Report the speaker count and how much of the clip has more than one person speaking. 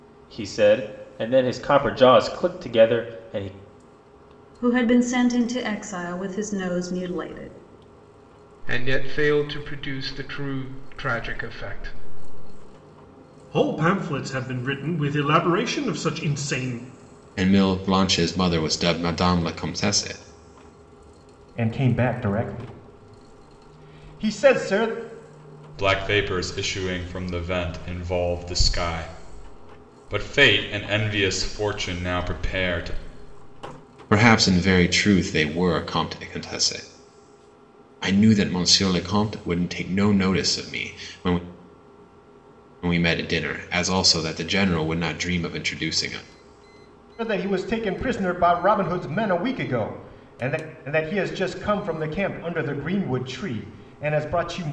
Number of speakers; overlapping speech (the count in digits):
7, no overlap